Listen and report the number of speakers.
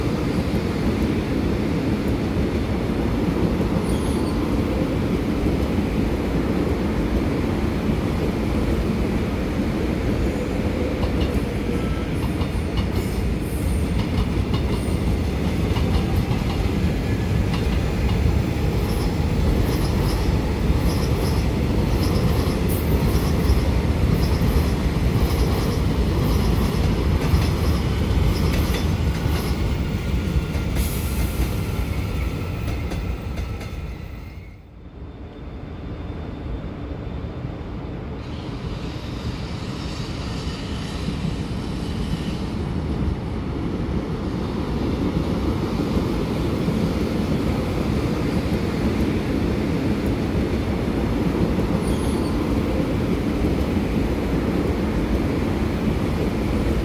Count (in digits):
0